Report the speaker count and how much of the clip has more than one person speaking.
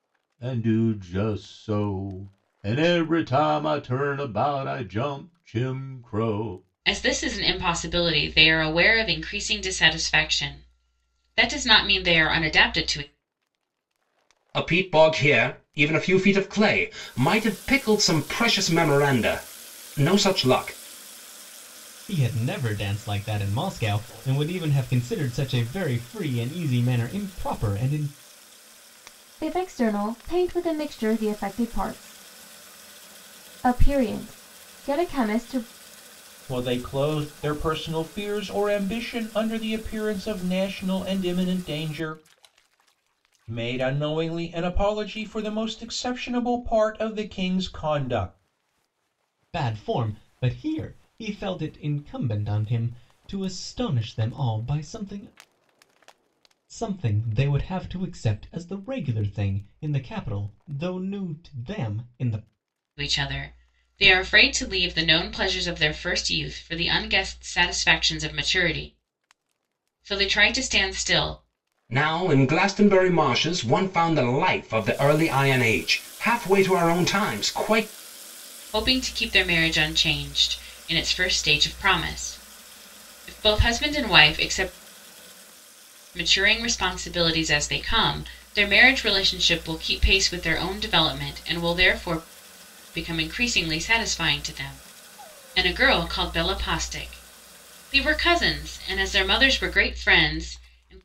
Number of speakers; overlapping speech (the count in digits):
6, no overlap